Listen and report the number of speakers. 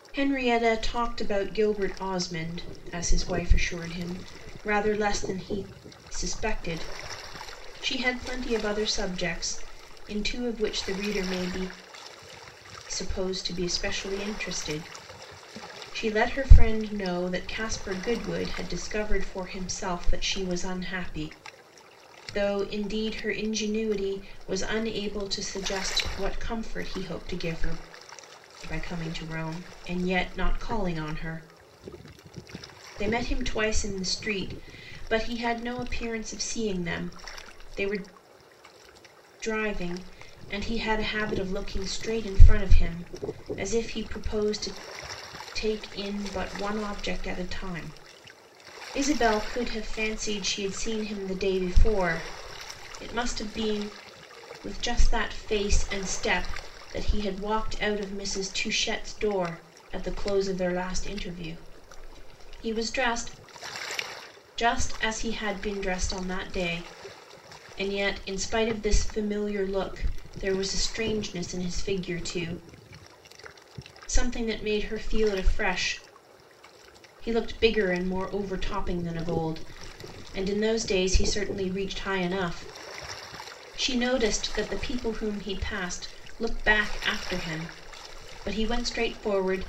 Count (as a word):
one